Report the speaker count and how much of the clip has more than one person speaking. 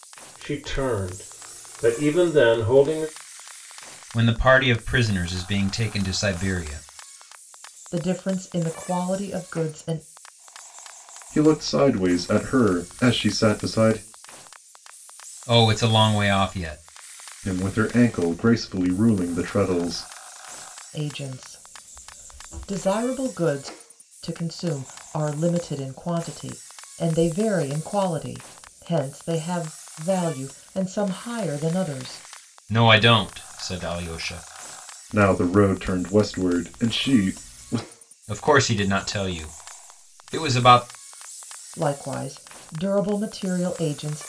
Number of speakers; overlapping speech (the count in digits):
4, no overlap